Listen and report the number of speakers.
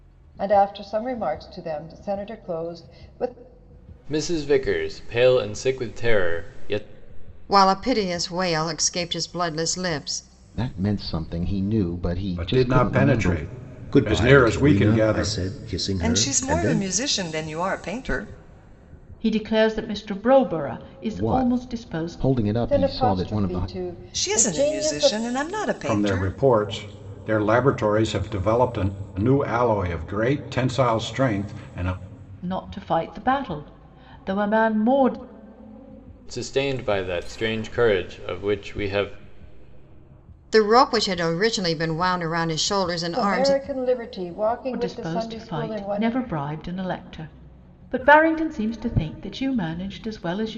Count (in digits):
8